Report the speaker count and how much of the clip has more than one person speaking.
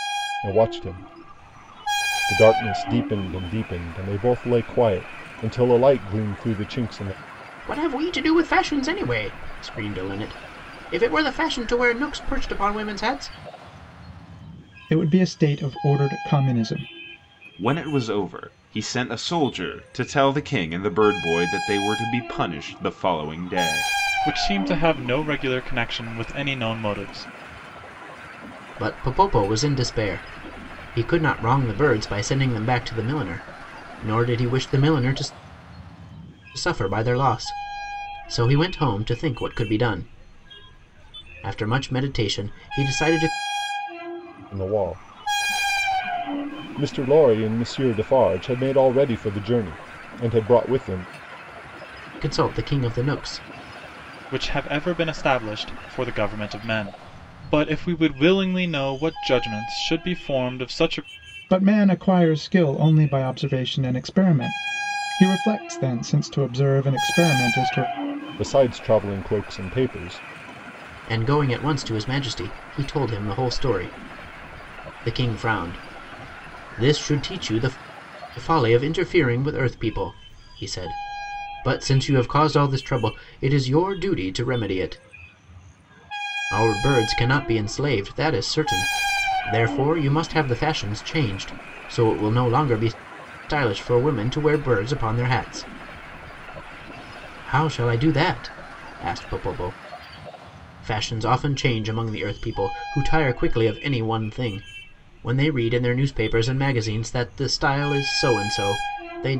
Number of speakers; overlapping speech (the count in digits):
5, no overlap